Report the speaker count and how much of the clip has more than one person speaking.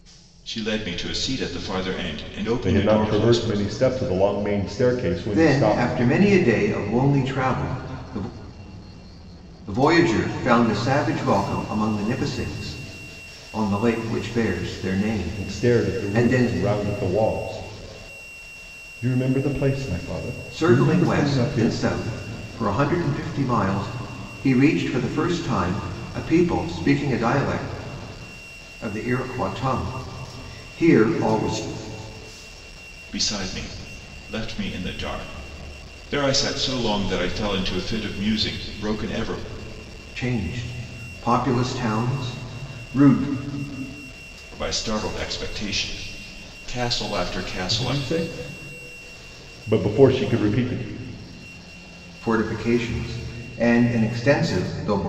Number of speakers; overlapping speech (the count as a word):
three, about 8%